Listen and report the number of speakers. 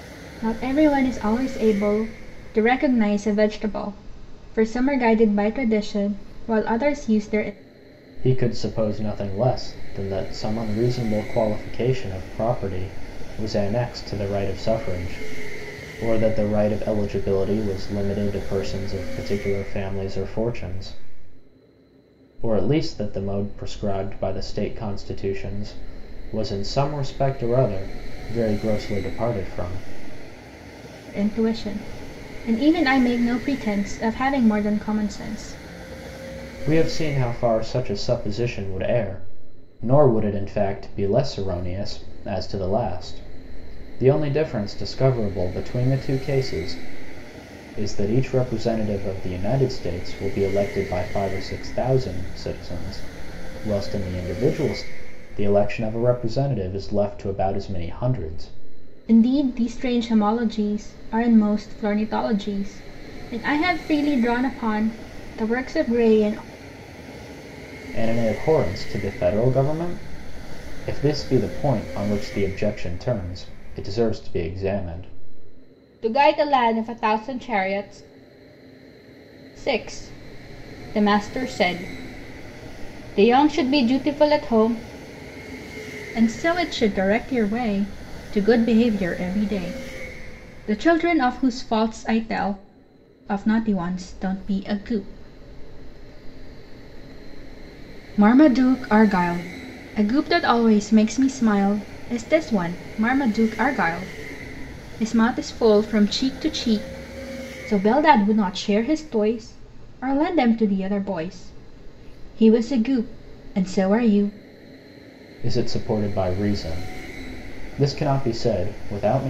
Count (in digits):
2